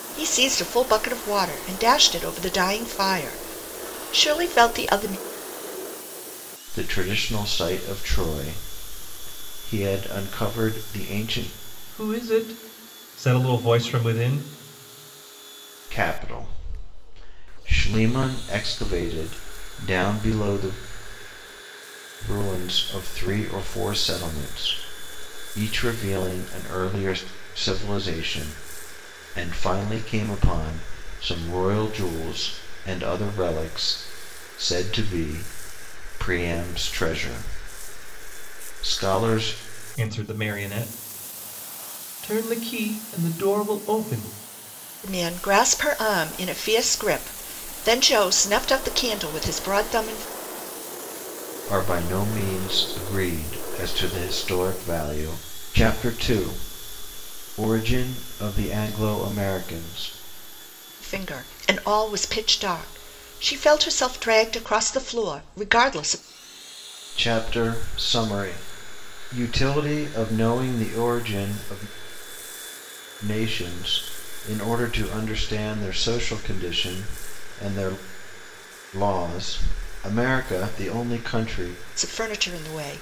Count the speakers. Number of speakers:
three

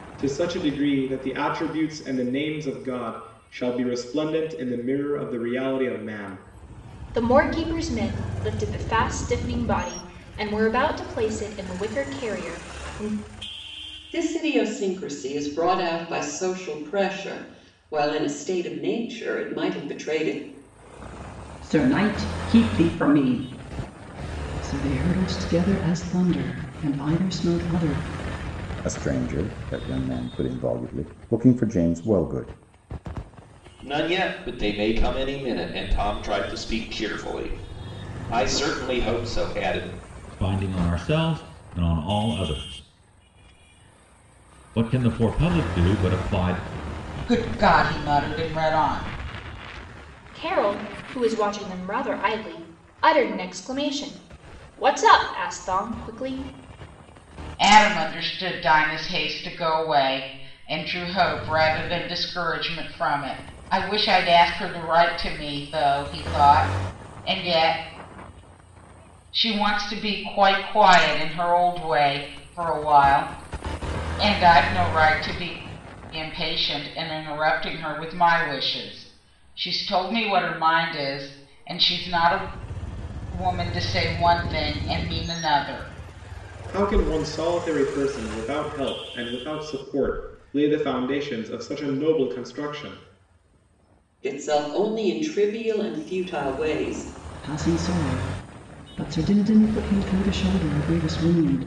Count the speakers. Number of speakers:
eight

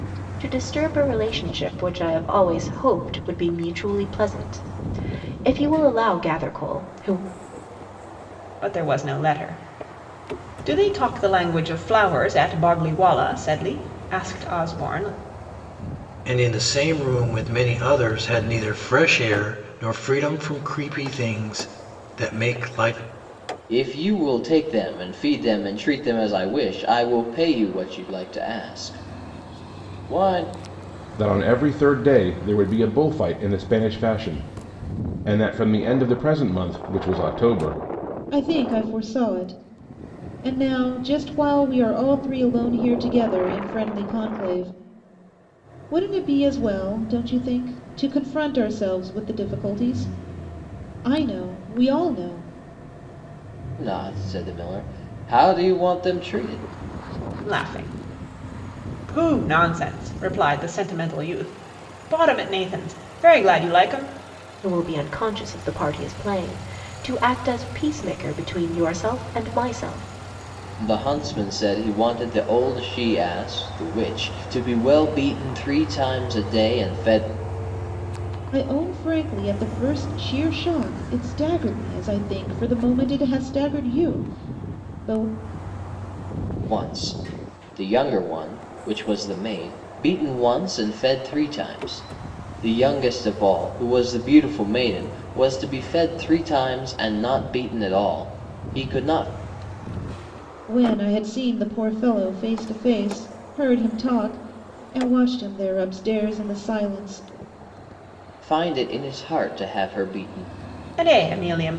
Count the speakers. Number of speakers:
six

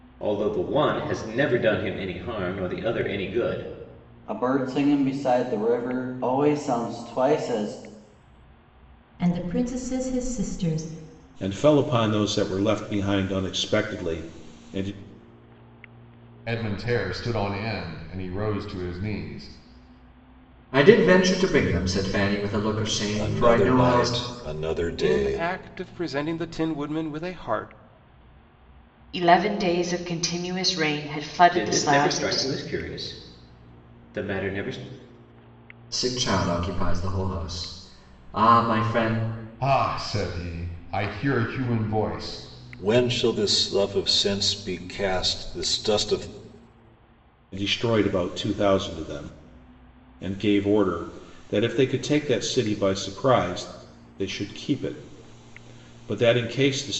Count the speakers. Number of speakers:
nine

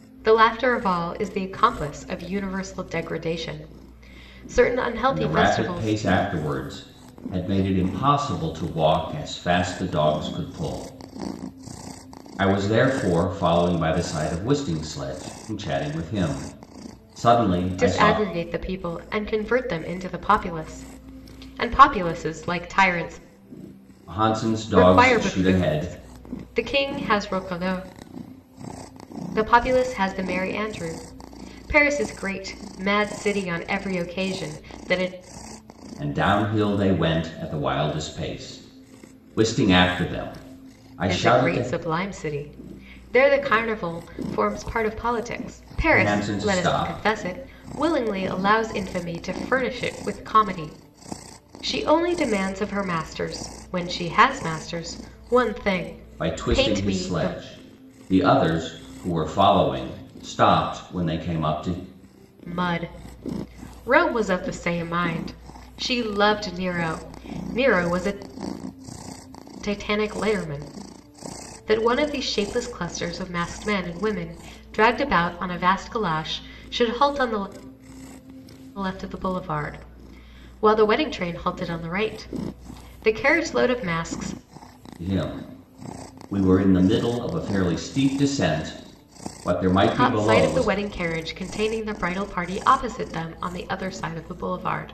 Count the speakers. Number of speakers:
two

